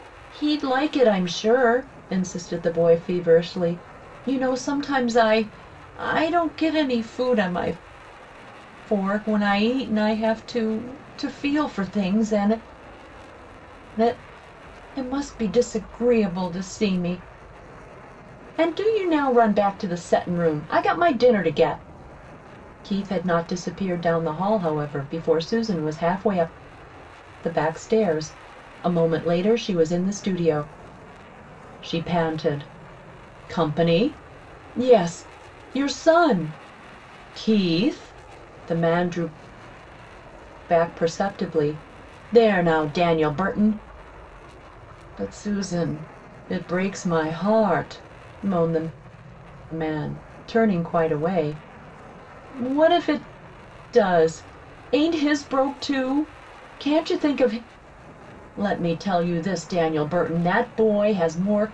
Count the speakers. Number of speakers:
1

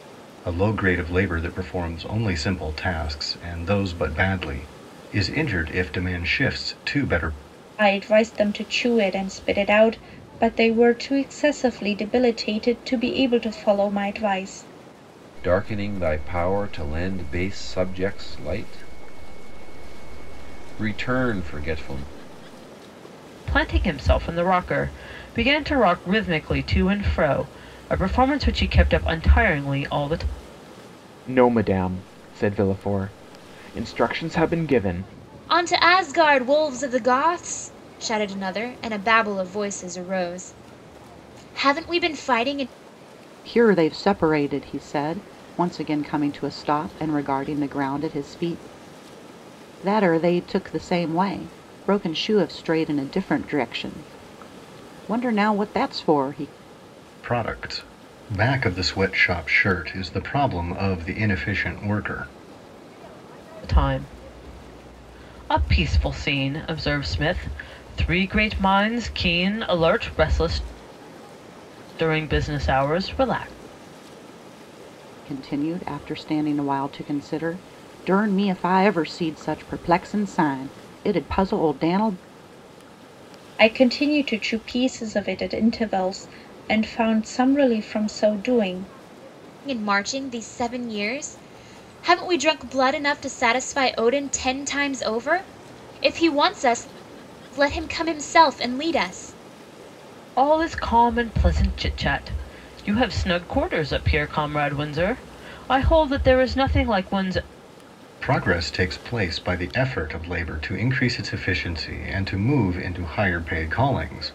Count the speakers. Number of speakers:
7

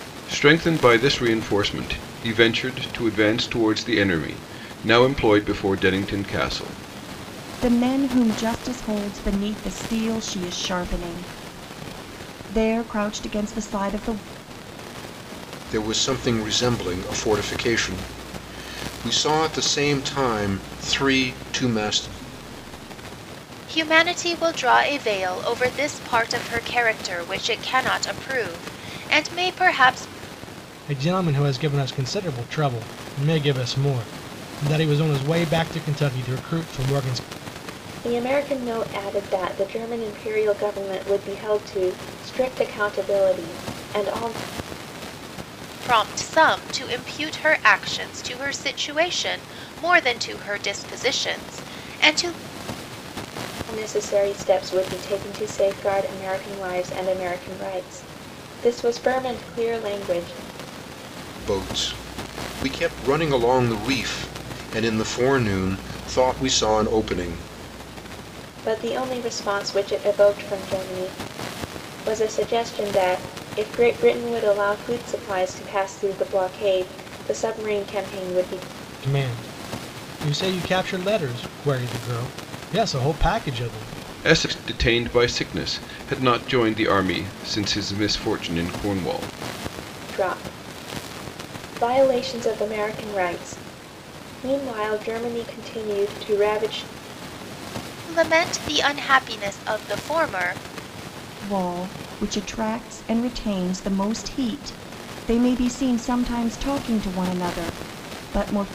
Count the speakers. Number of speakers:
6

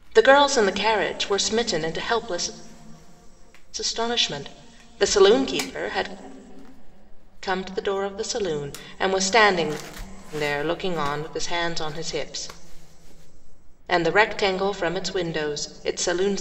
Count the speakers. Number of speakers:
1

